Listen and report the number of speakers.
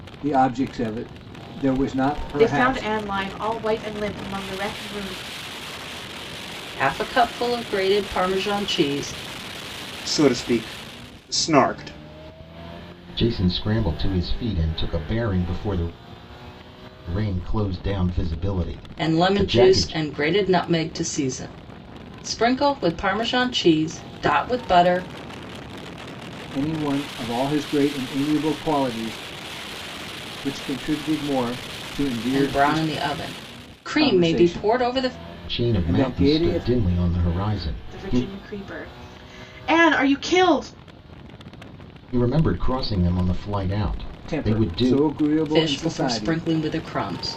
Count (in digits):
5